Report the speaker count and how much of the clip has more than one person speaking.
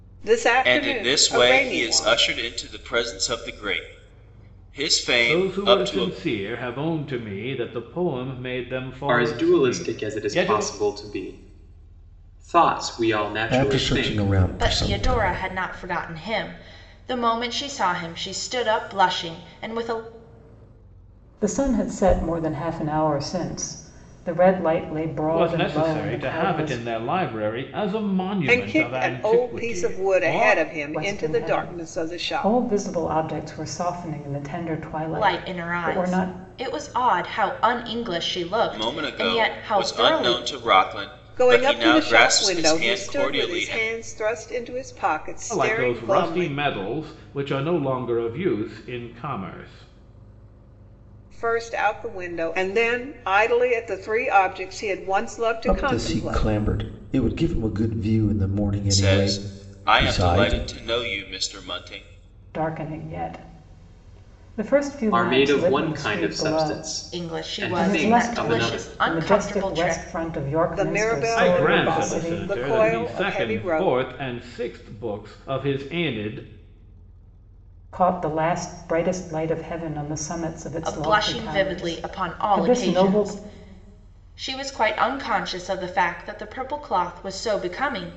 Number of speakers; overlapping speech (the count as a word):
seven, about 36%